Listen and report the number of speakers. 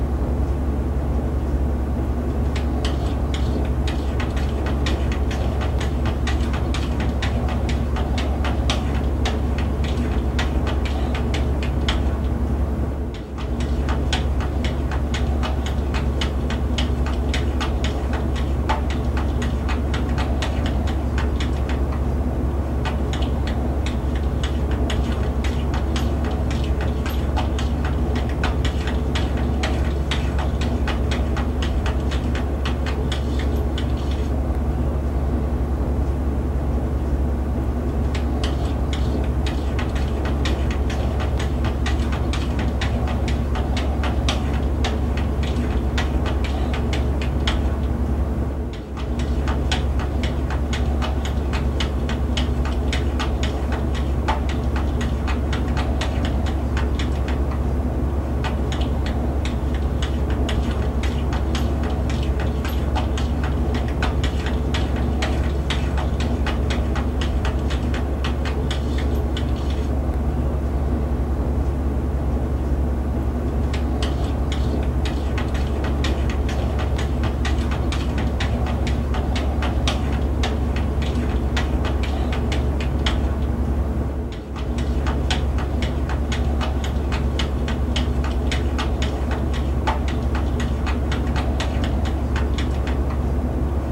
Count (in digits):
0